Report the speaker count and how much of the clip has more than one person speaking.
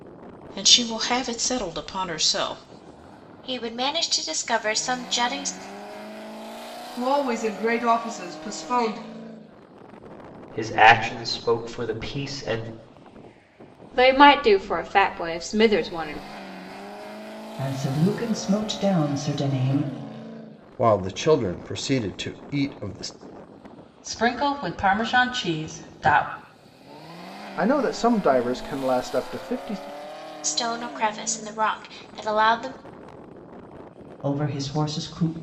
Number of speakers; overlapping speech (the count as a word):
nine, no overlap